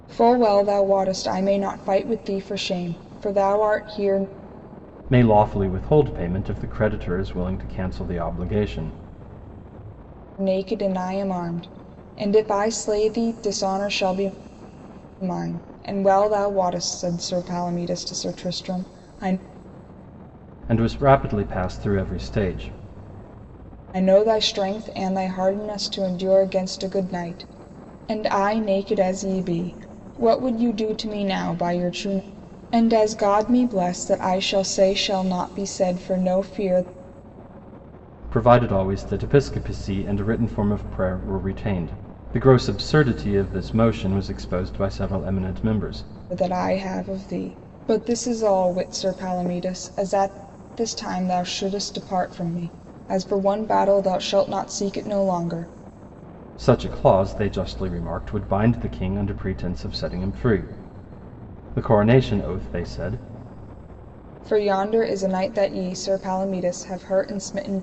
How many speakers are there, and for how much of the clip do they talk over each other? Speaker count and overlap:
two, no overlap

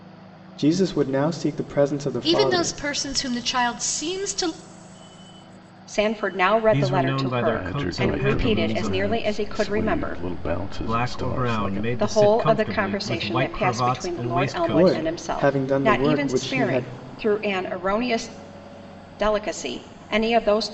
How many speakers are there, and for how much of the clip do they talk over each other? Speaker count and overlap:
five, about 49%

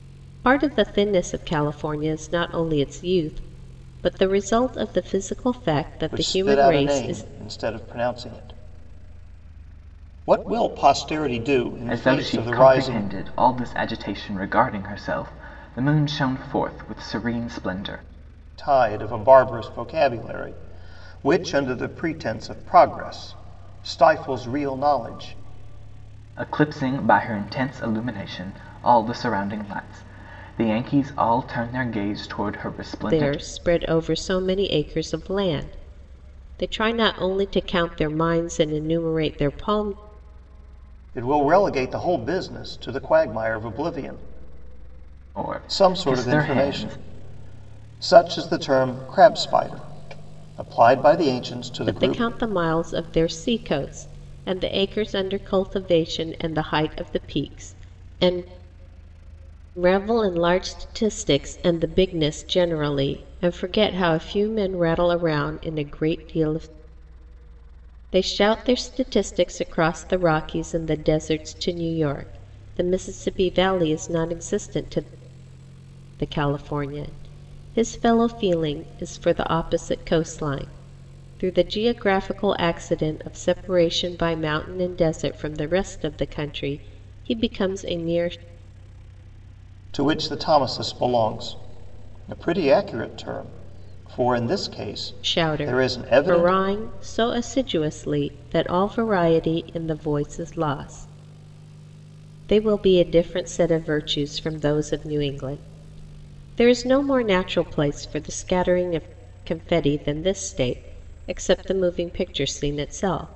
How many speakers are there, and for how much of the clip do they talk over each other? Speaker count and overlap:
three, about 5%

